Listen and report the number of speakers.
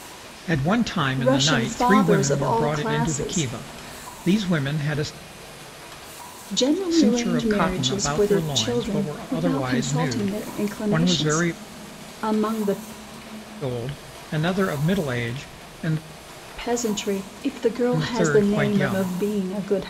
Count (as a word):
two